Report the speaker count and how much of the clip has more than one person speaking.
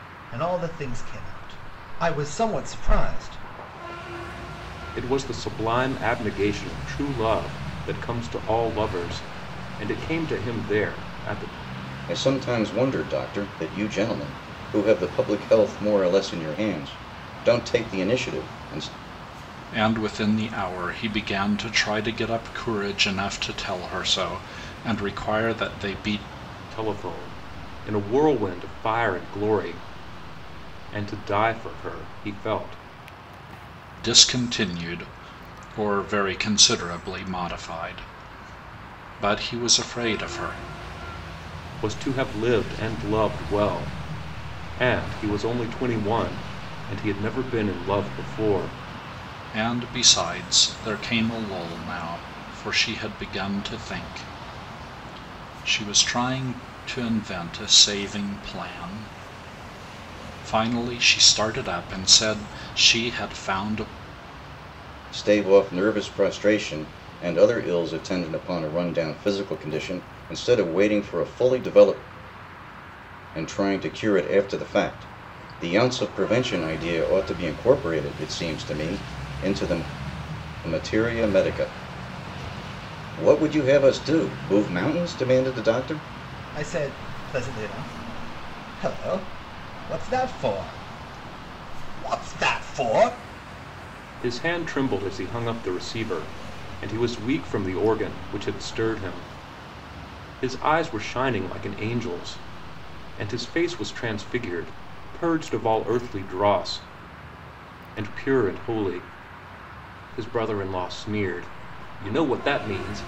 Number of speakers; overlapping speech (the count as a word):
four, no overlap